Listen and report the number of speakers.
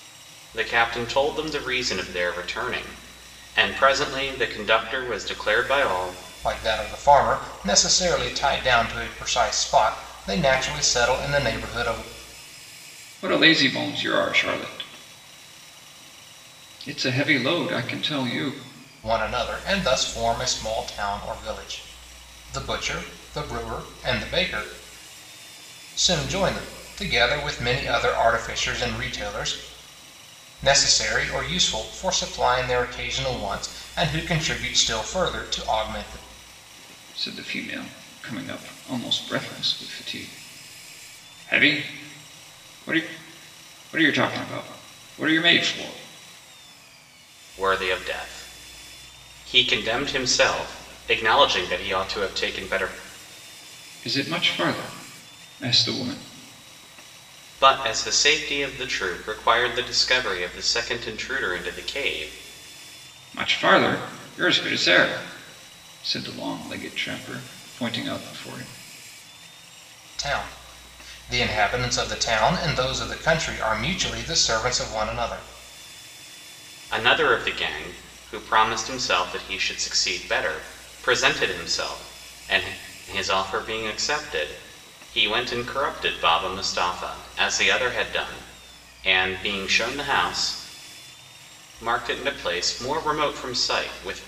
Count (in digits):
3